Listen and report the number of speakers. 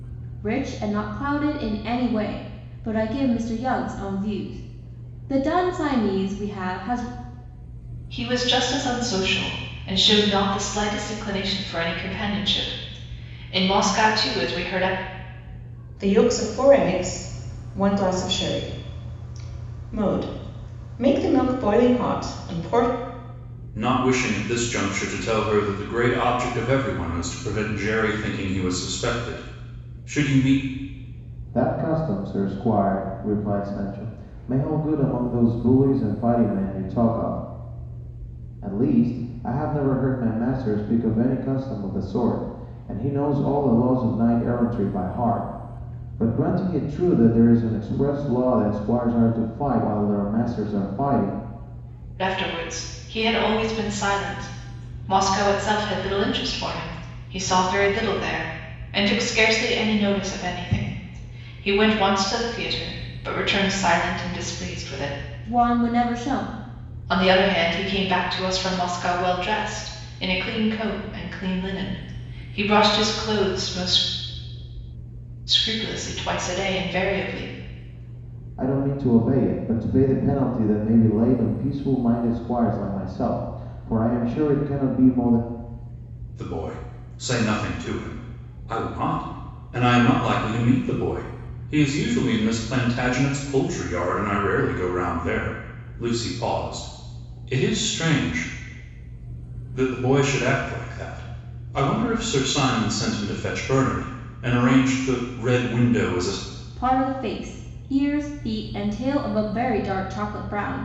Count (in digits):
5